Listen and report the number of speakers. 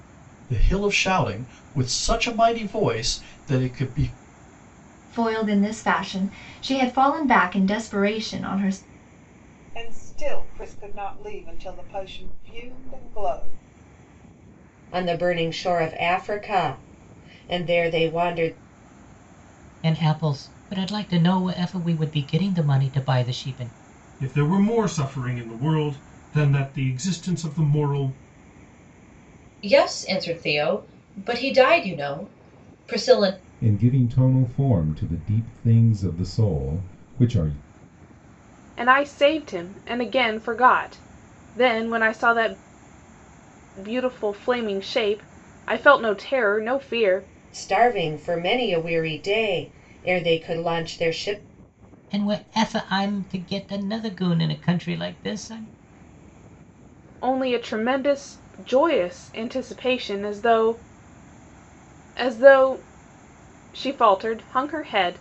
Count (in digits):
9